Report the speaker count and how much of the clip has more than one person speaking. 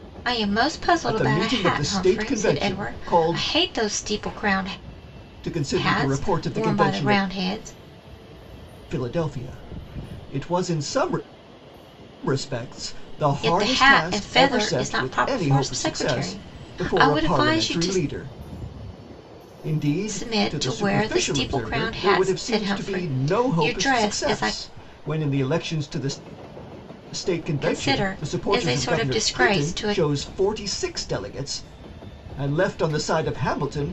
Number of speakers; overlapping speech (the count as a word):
two, about 45%